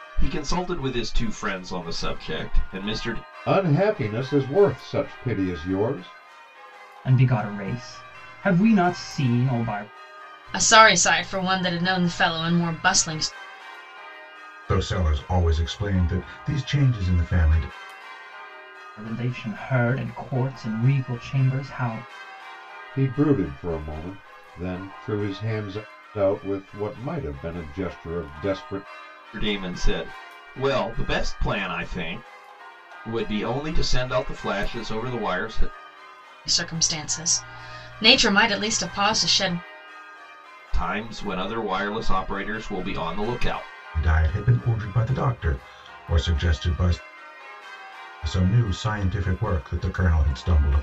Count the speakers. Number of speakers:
five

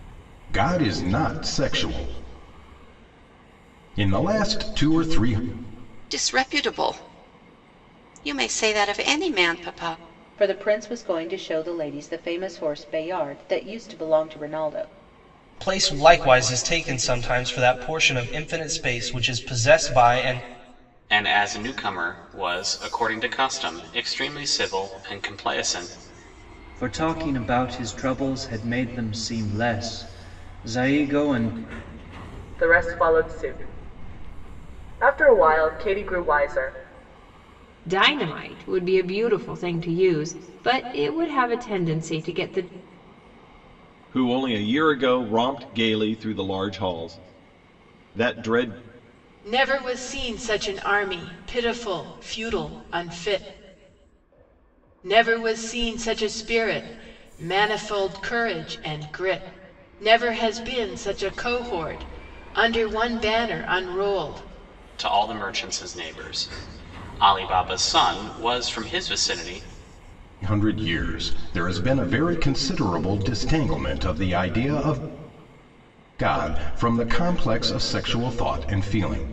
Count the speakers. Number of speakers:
ten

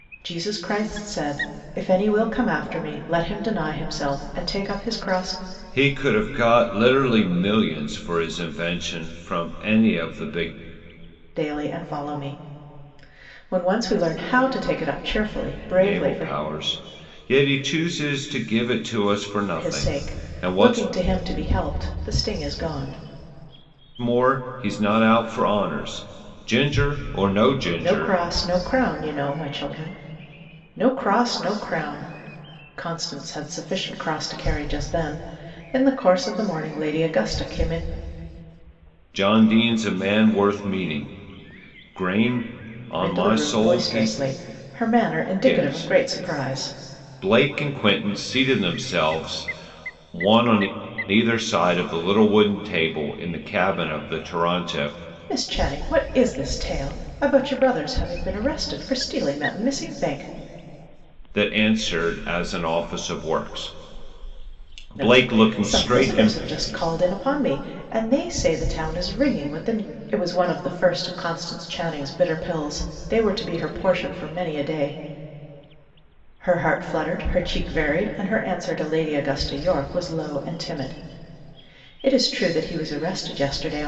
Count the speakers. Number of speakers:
two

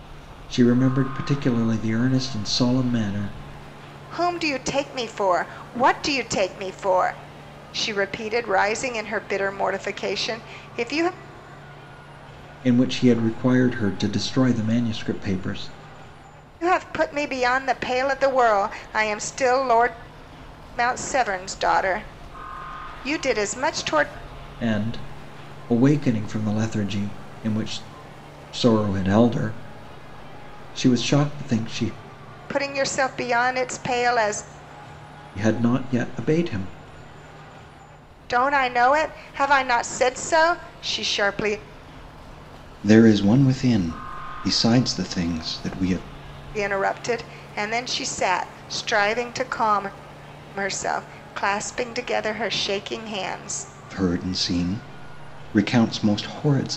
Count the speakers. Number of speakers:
two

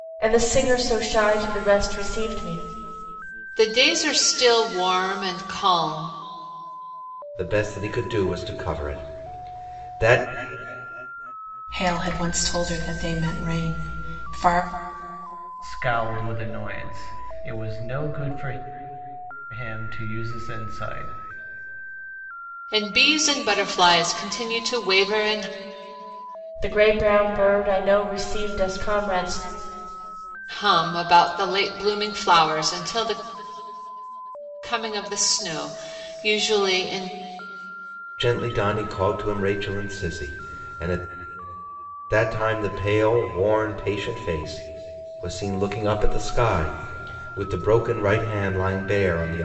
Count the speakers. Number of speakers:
five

